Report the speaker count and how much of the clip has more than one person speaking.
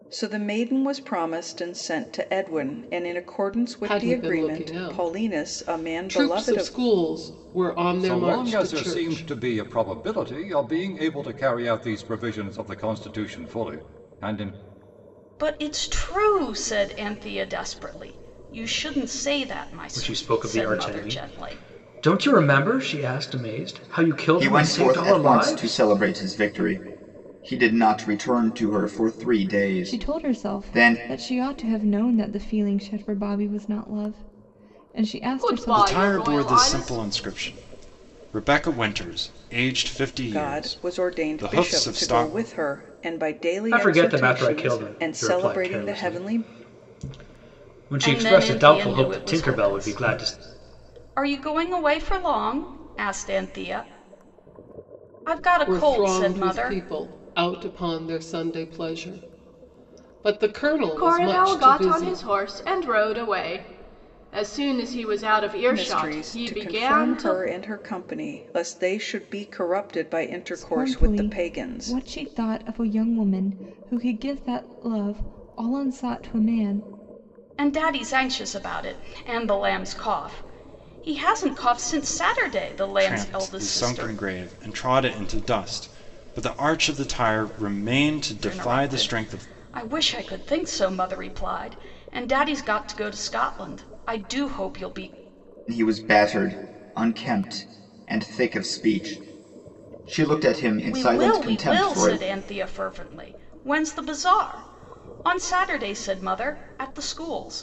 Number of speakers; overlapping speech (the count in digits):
9, about 25%